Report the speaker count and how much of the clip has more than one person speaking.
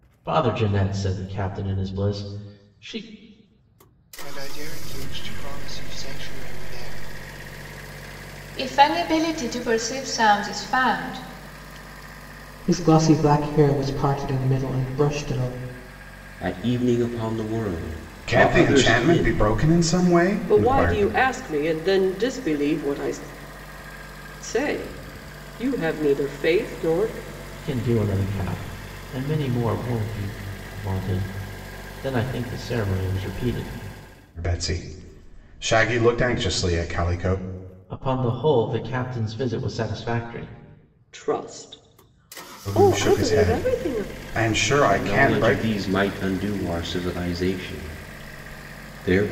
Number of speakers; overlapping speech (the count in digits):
7, about 8%